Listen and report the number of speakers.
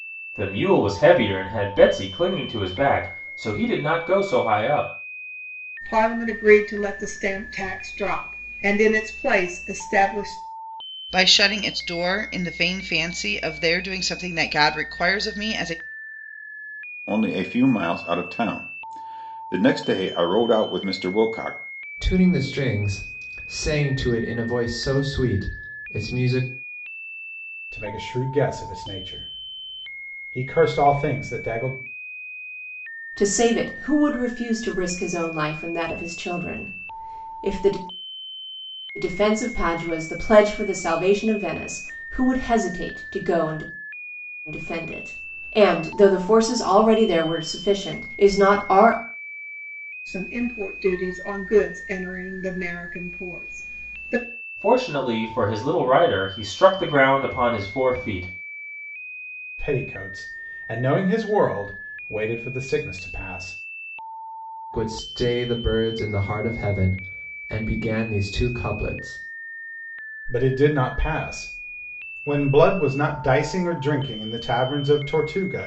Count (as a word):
seven